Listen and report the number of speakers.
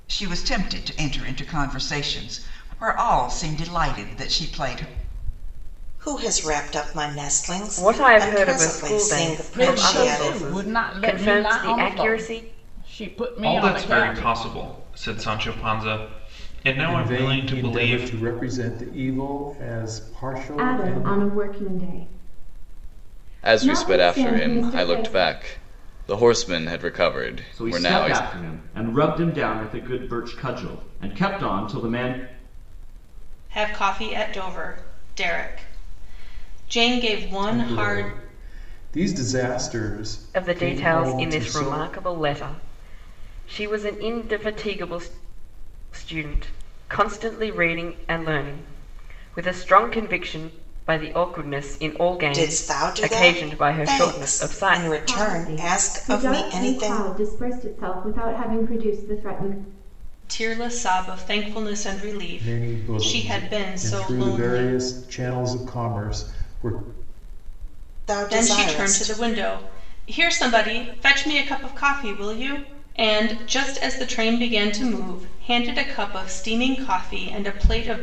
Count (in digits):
10